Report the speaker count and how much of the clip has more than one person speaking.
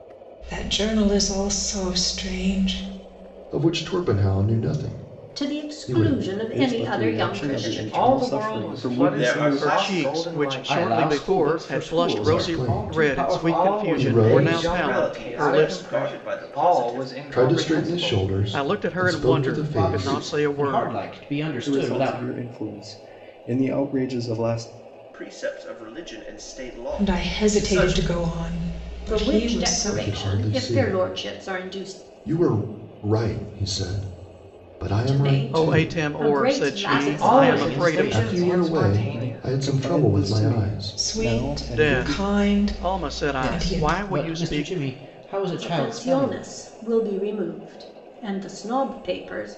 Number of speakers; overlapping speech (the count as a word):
eight, about 61%